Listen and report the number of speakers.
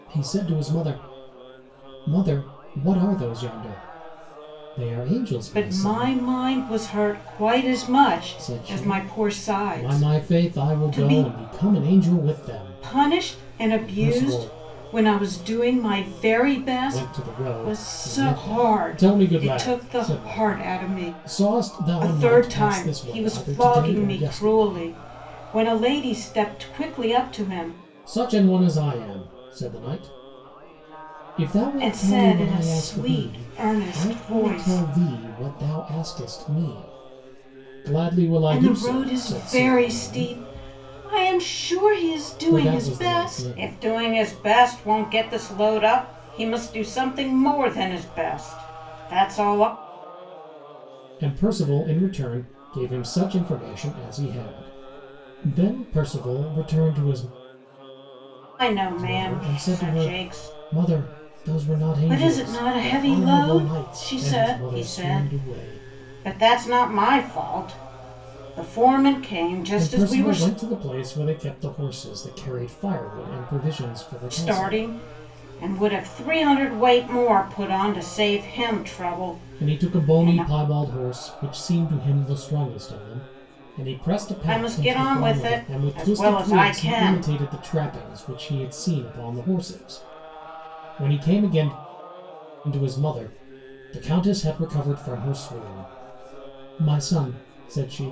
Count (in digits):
2